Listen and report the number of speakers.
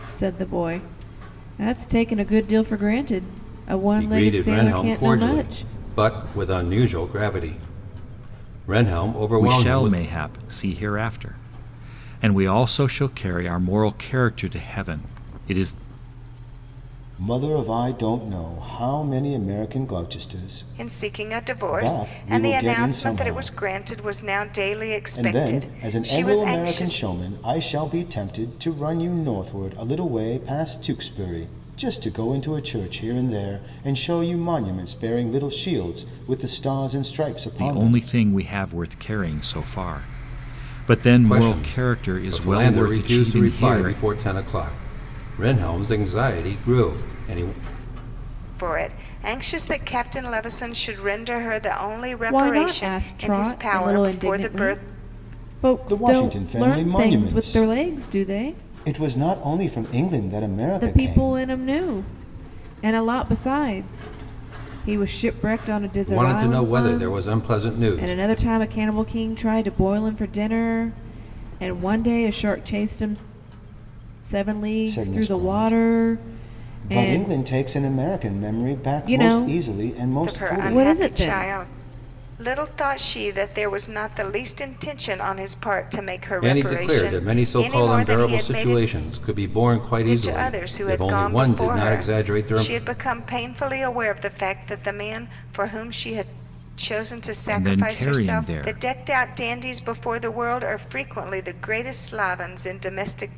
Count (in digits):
5